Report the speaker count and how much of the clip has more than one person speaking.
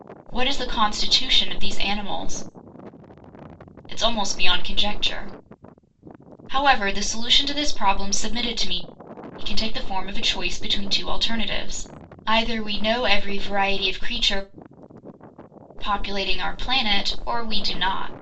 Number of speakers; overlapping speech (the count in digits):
1, no overlap